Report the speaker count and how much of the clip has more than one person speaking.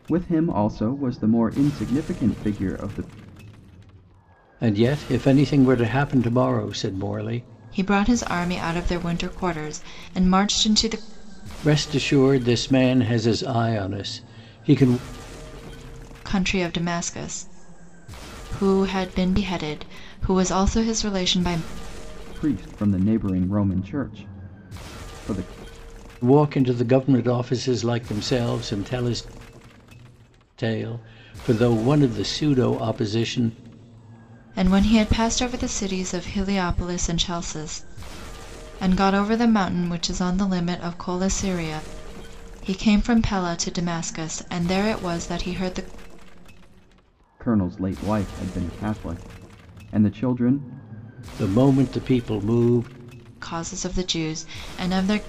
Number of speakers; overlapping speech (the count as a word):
three, no overlap